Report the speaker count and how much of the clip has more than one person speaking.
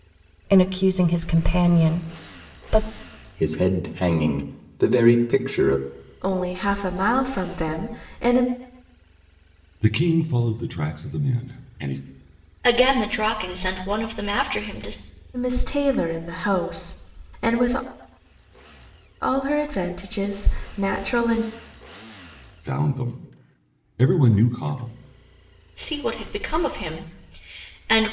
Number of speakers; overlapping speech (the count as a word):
five, no overlap